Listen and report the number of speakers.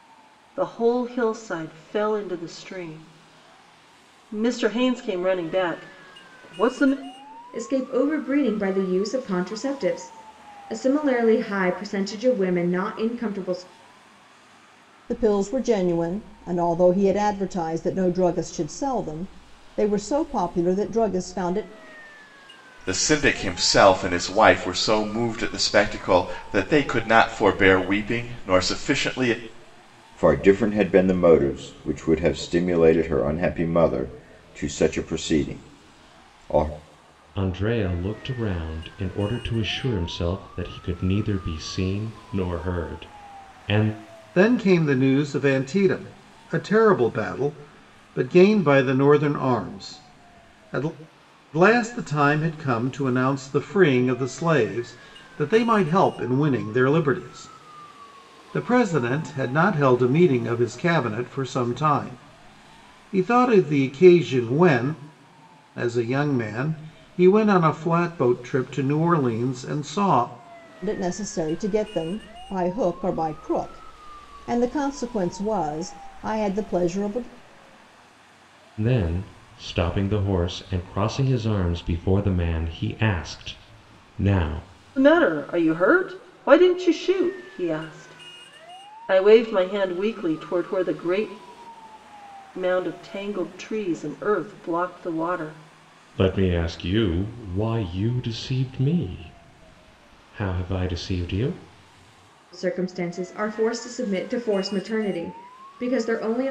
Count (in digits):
7